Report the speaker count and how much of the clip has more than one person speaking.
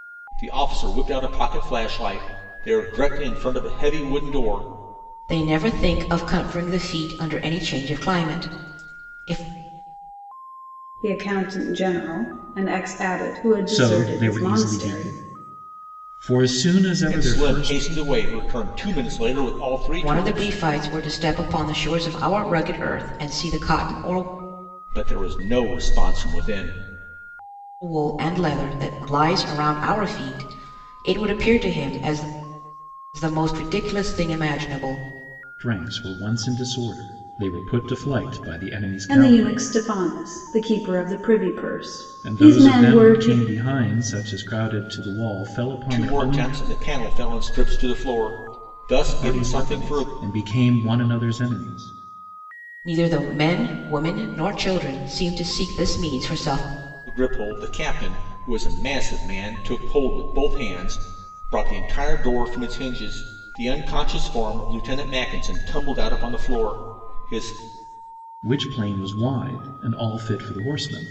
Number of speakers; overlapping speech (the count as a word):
four, about 9%